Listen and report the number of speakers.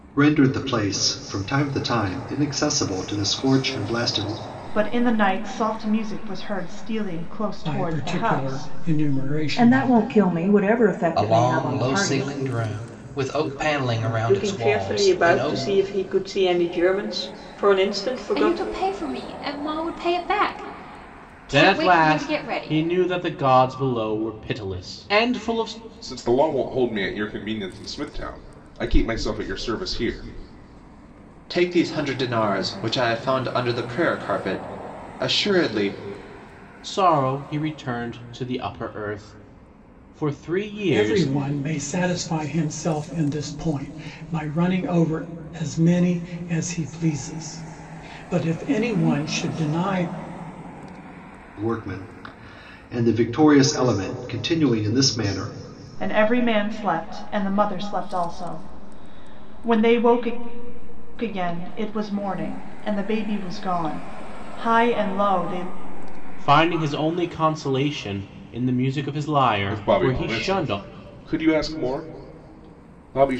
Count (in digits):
10